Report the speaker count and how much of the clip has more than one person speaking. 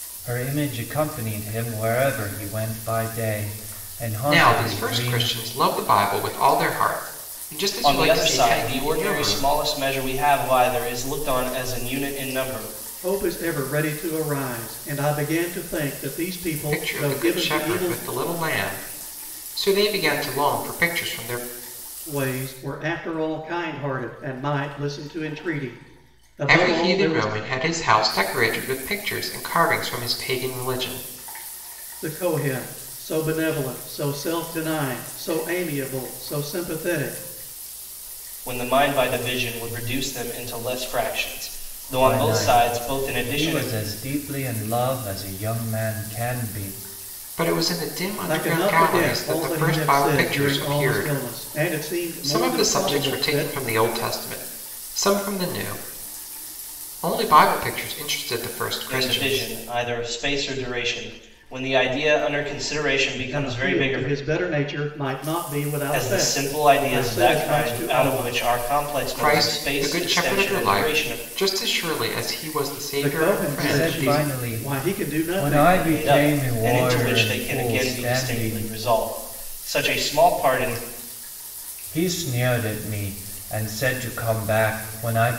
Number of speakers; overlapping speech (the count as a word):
four, about 27%